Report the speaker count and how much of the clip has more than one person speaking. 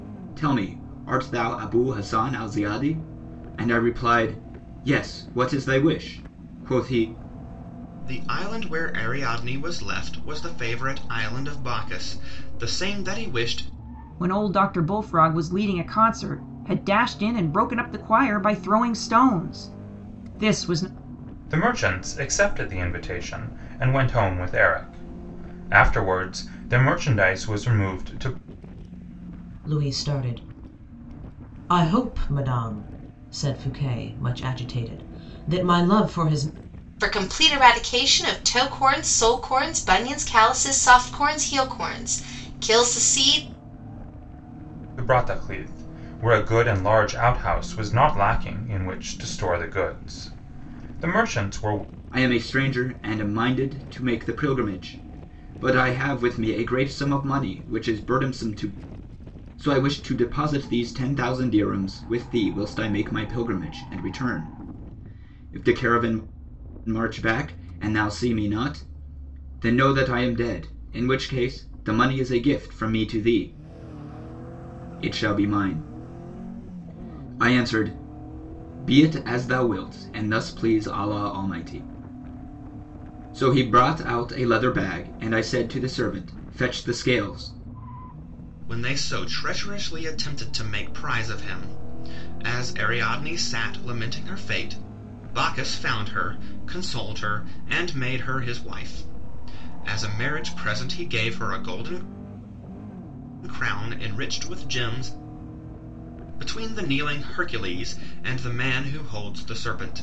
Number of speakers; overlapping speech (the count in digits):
6, no overlap